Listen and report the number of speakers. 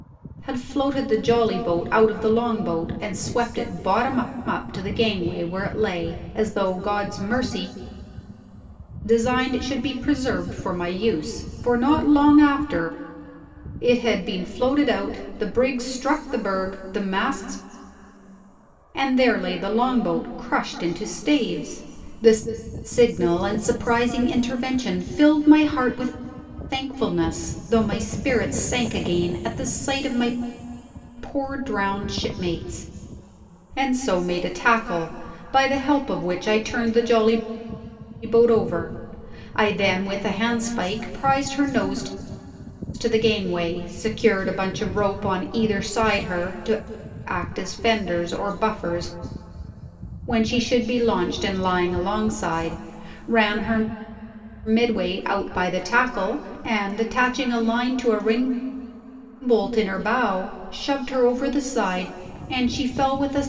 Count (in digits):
1